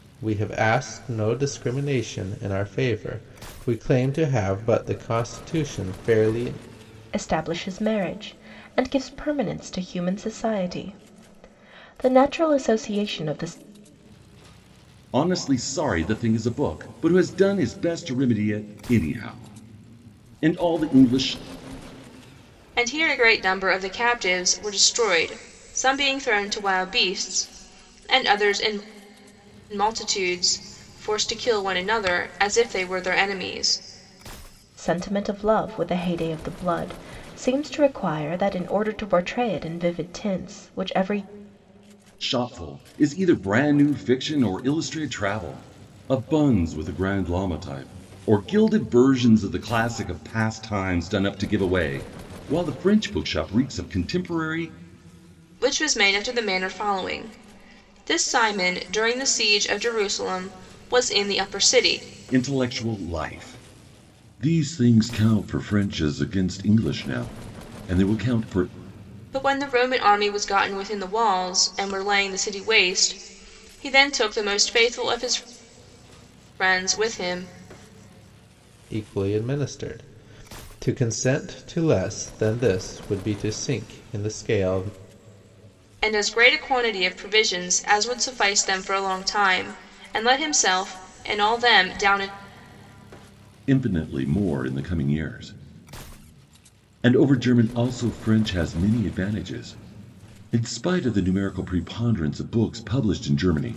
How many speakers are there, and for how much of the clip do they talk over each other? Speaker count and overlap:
four, no overlap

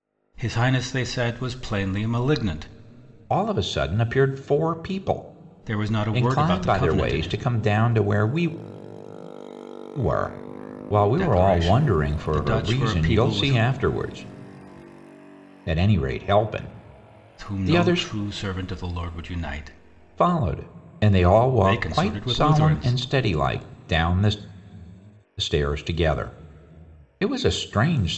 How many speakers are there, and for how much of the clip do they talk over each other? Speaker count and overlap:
two, about 21%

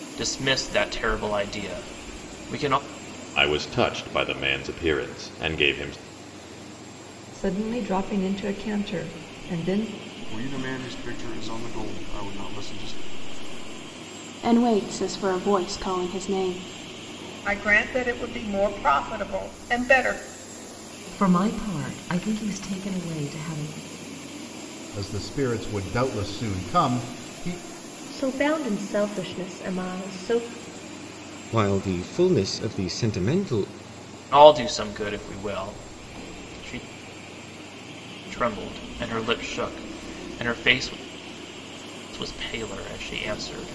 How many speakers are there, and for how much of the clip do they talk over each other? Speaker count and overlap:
ten, no overlap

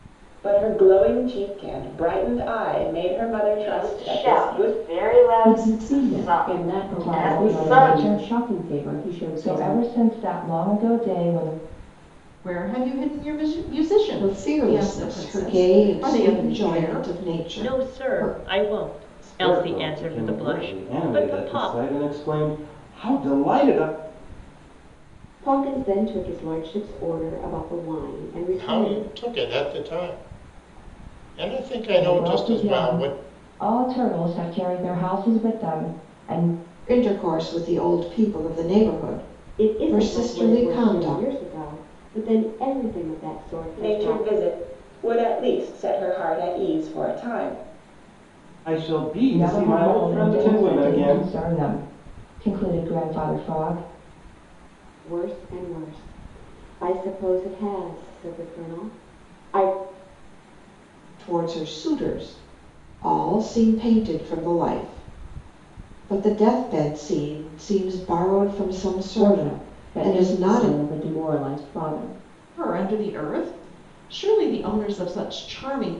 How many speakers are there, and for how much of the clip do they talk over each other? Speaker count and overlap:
ten, about 26%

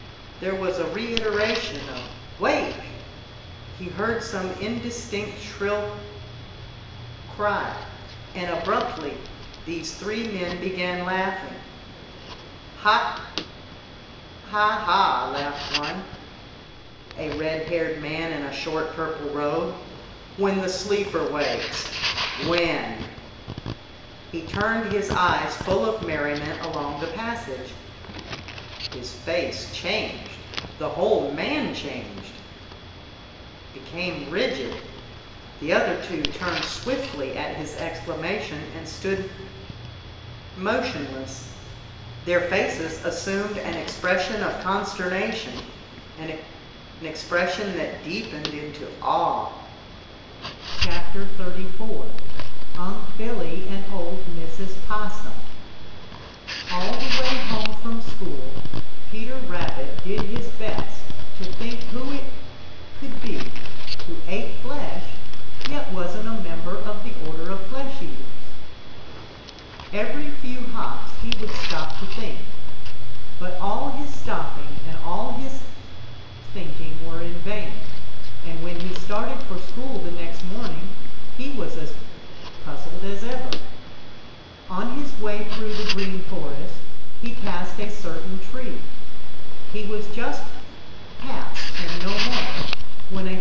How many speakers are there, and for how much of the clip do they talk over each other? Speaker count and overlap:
one, no overlap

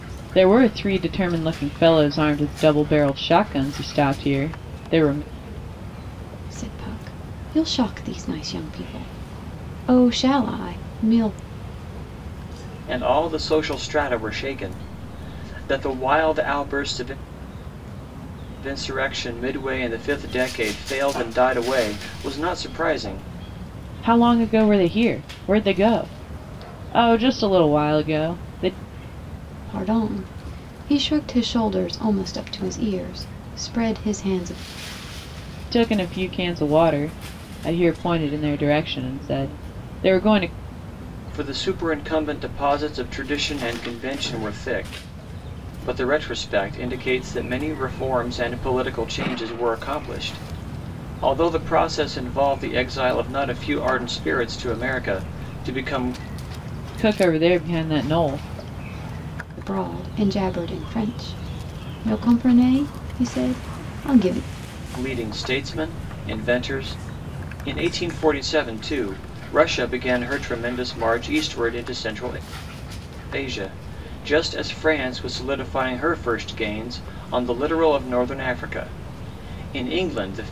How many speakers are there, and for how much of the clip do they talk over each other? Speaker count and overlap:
three, no overlap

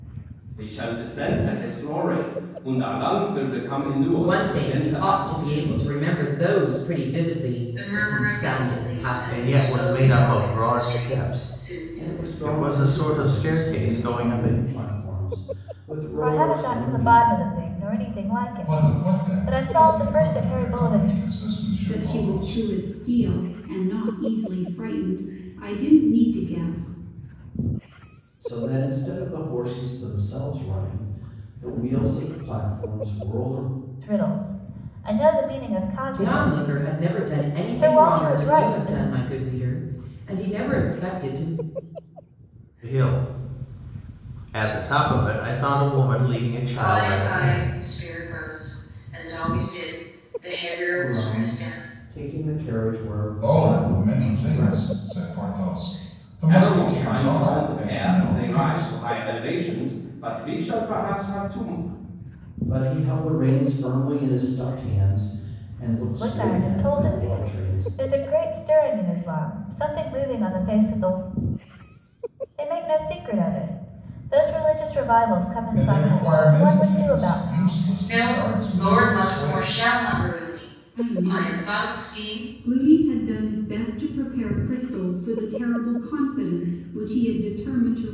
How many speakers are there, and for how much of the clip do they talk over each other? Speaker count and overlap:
eight, about 33%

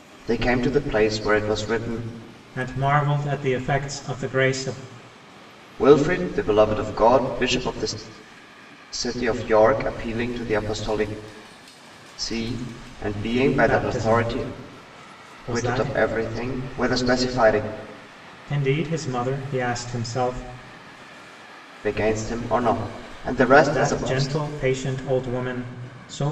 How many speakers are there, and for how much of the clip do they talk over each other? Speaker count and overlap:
two, about 8%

